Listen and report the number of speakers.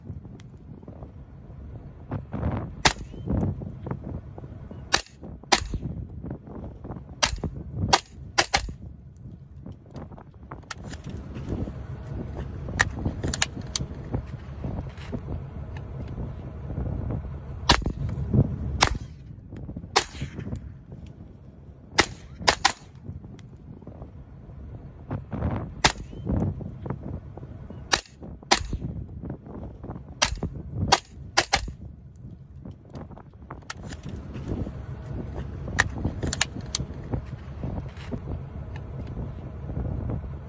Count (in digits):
0